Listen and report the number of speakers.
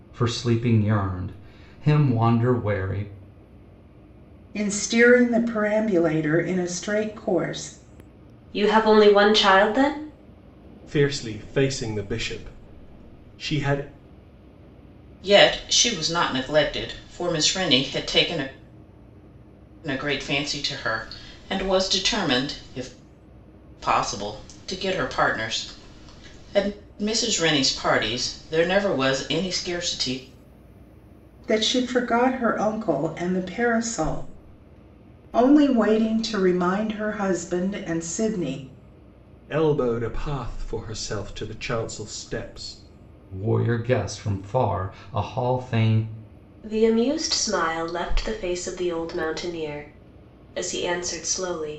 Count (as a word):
five